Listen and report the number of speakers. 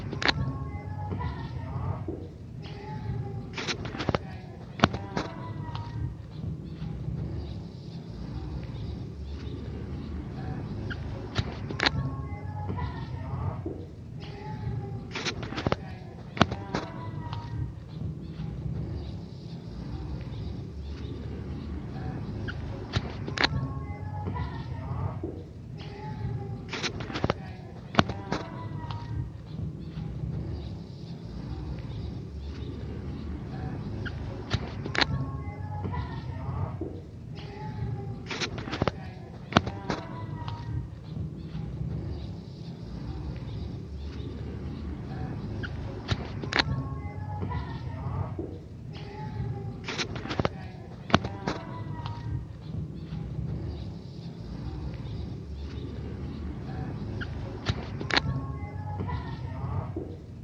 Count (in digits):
0